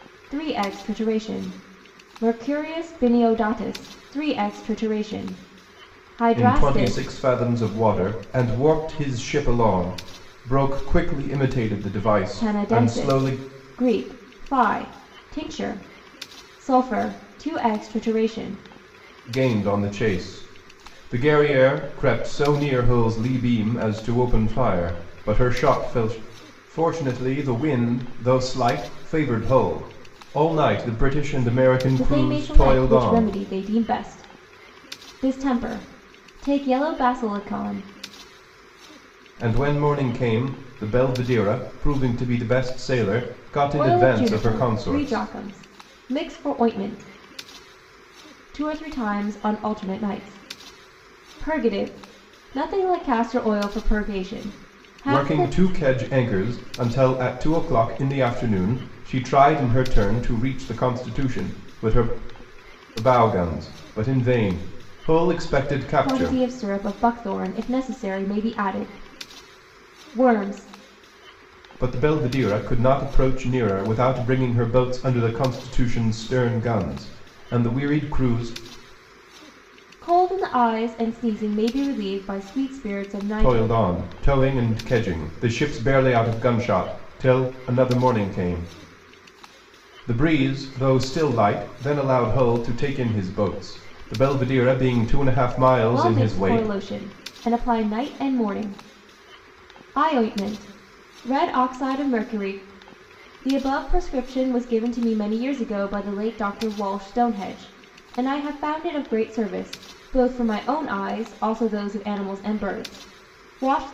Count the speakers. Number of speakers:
2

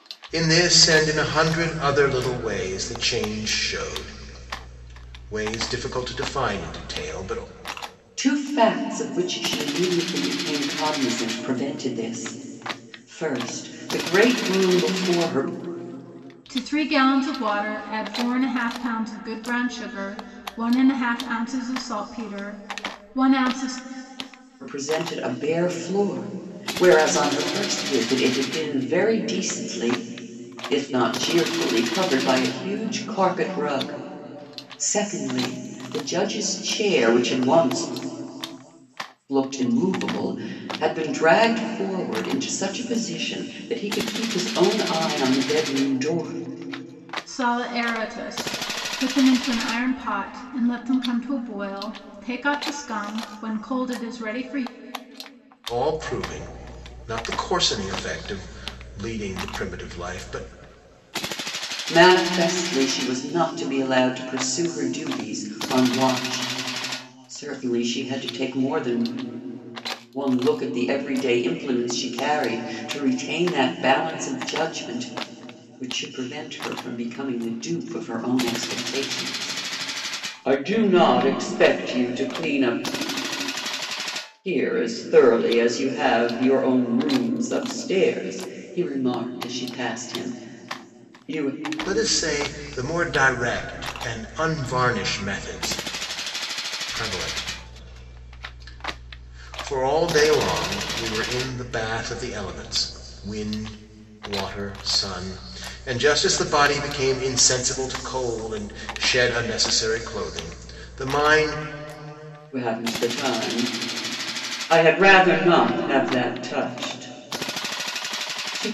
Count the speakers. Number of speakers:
3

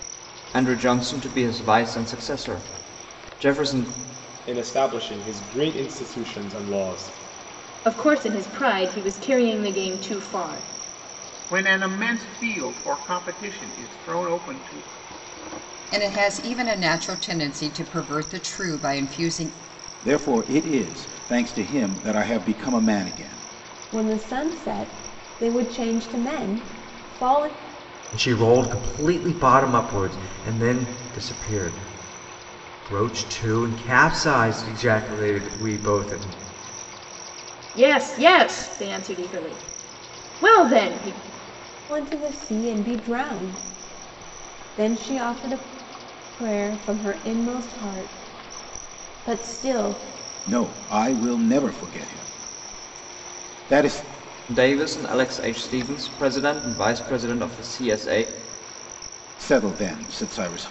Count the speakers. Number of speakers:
8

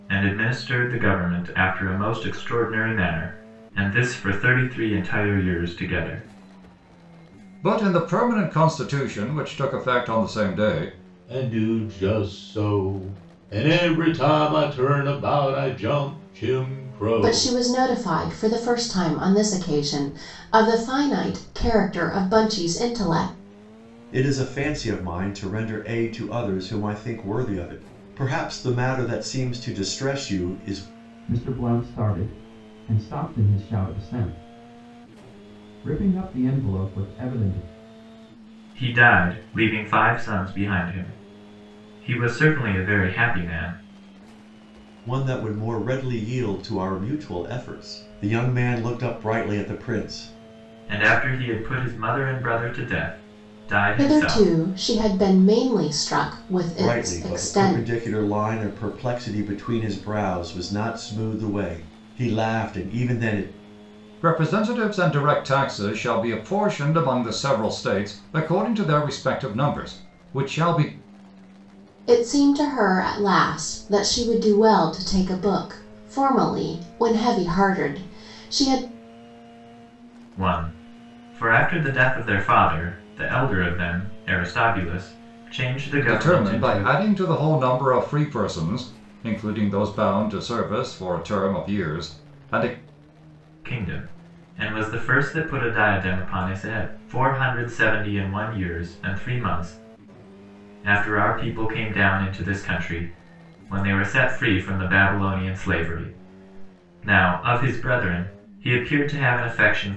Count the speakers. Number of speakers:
6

